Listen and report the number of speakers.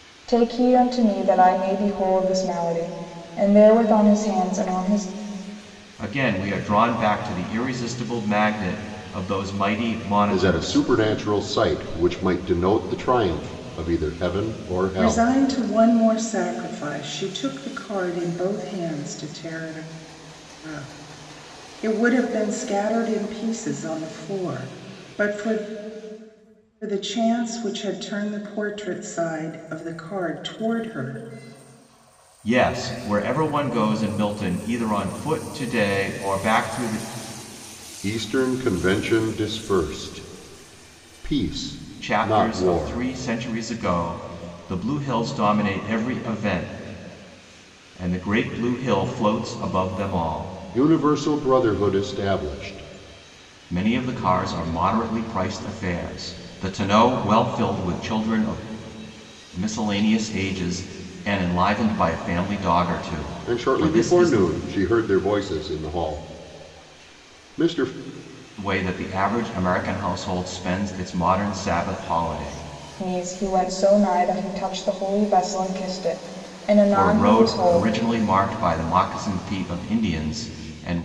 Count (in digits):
4